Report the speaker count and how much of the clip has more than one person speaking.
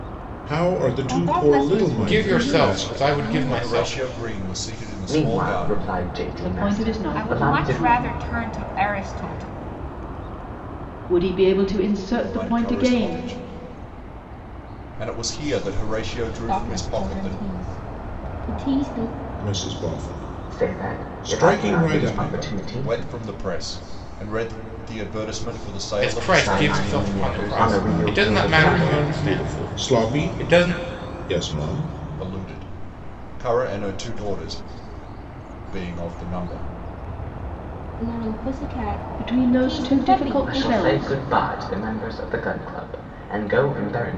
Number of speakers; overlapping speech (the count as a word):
seven, about 39%